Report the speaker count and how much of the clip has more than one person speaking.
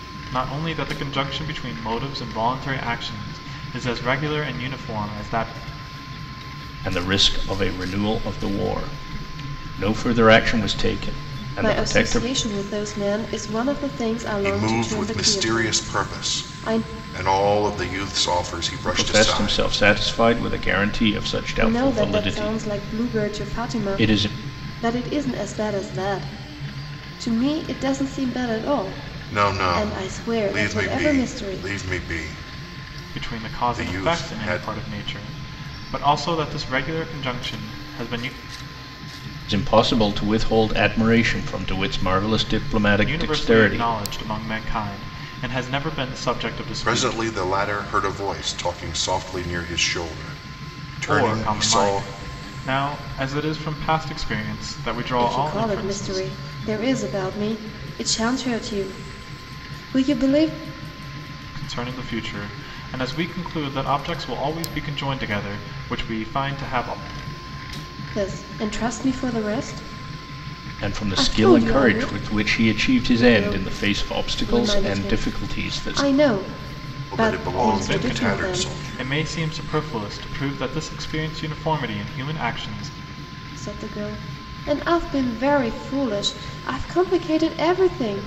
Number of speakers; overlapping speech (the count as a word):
four, about 23%